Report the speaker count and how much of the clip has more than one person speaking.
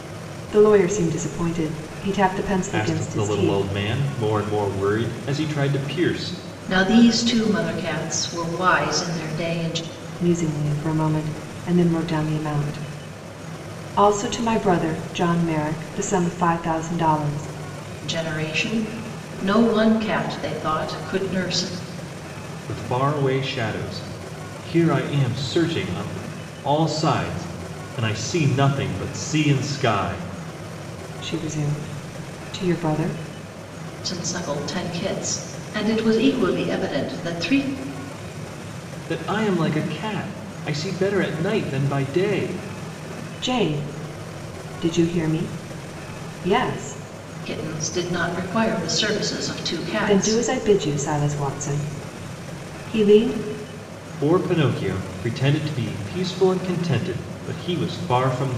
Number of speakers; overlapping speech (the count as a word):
three, about 2%